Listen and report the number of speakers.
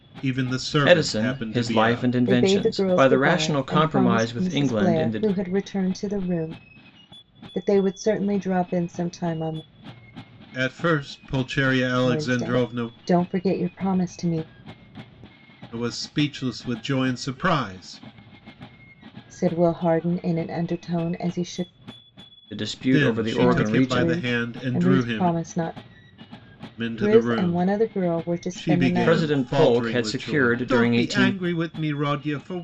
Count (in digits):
3